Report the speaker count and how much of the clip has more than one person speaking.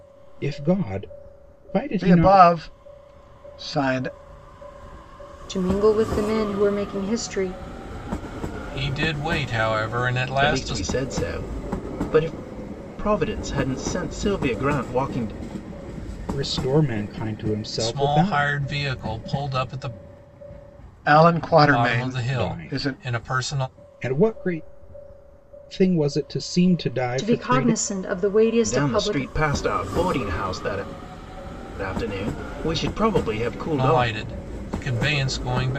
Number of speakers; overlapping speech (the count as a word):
five, about 15%